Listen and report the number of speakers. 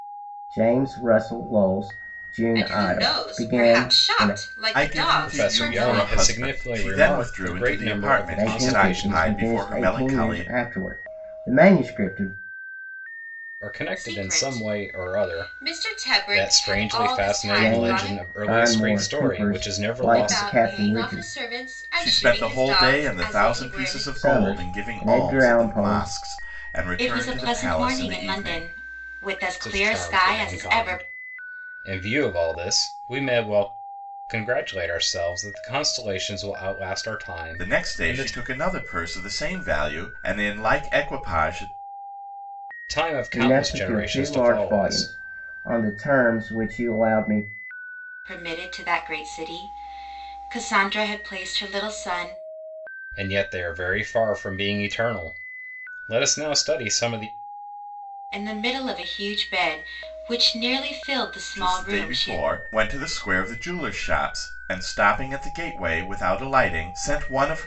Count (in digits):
4